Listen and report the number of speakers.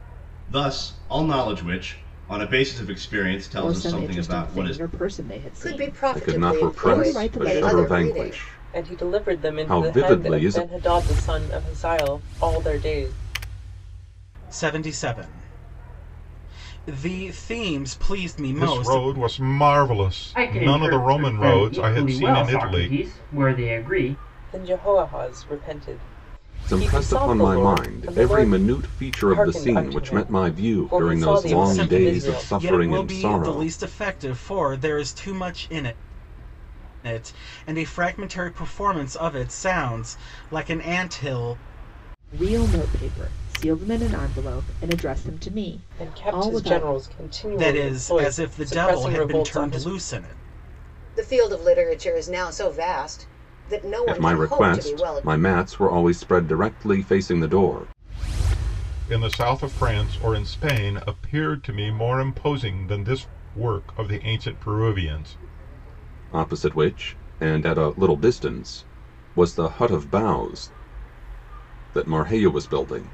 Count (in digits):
8